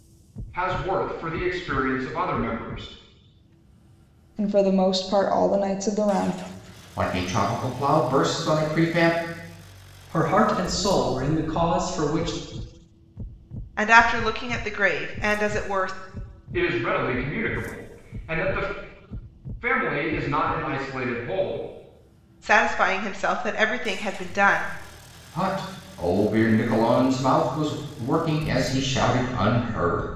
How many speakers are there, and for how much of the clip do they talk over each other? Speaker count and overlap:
five, no overlap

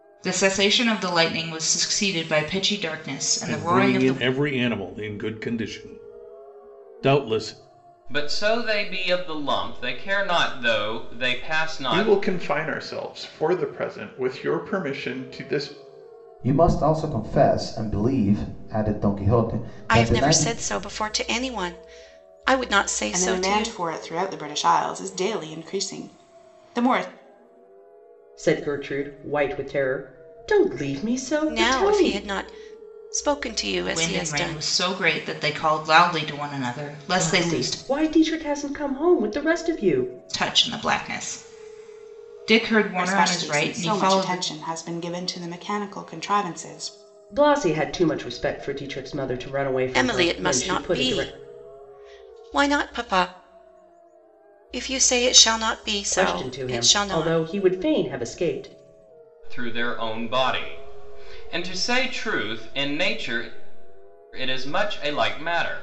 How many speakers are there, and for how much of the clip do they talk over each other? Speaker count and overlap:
eight, about 13%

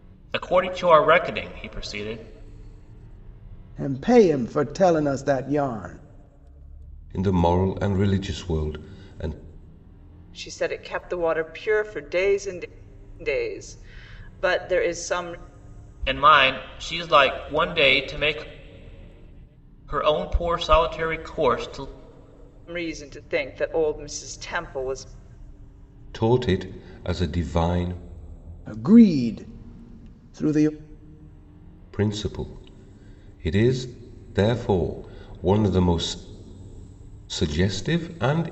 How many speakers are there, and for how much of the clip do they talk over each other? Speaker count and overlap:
four, no overlap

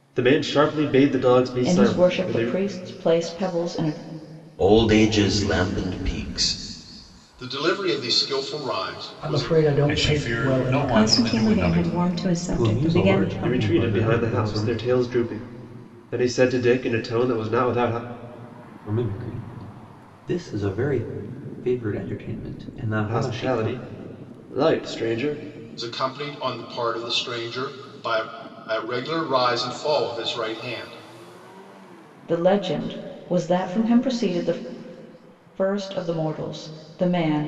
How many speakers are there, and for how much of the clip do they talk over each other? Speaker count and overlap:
eight, about 16%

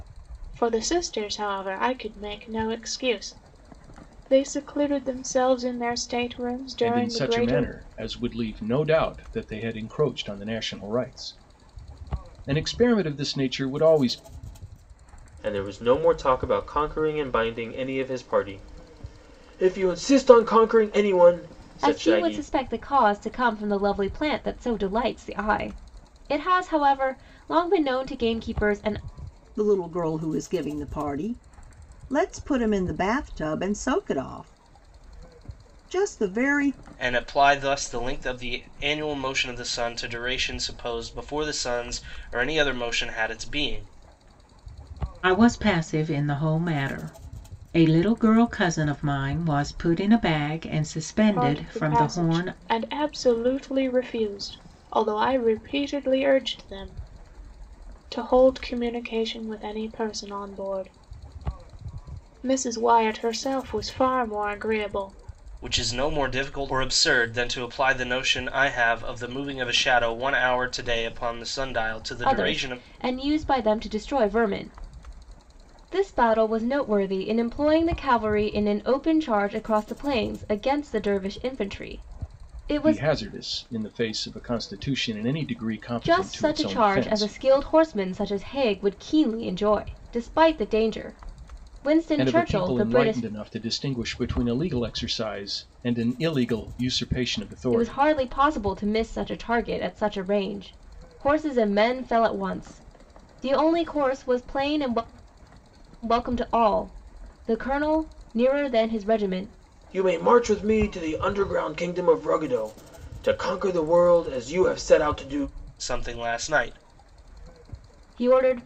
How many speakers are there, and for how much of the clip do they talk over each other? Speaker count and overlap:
seven, about 6%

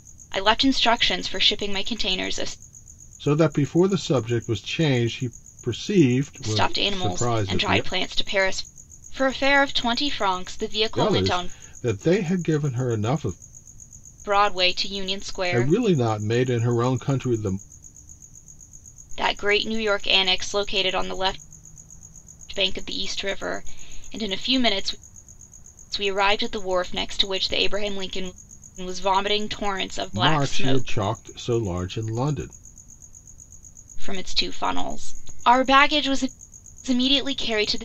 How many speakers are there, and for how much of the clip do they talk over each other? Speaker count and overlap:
two, about 8%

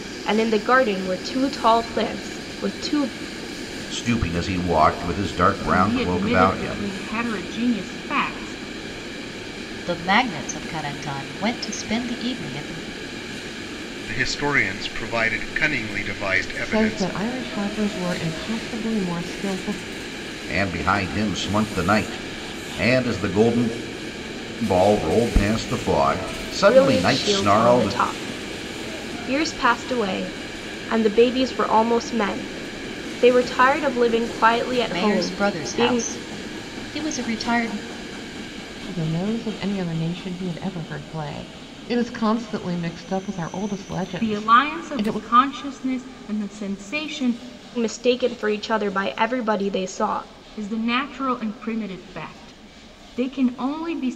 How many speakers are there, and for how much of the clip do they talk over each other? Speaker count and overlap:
six, about 10%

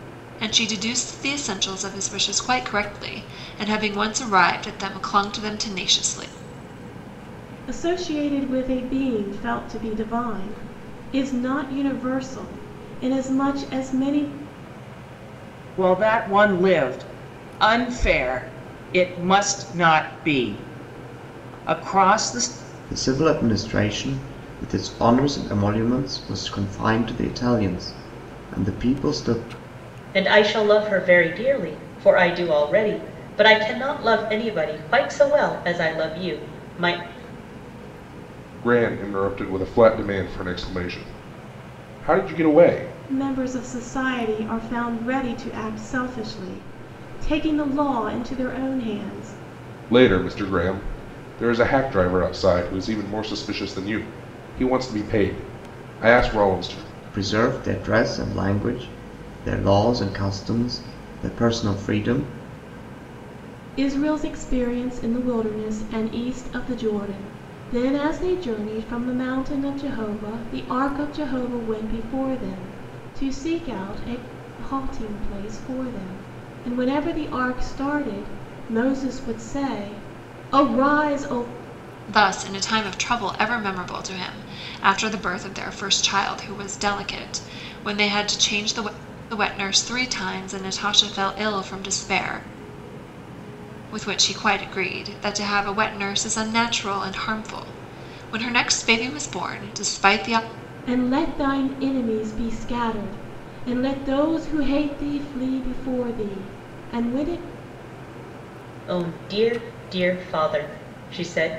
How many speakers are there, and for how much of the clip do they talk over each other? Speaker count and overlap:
six, no overlap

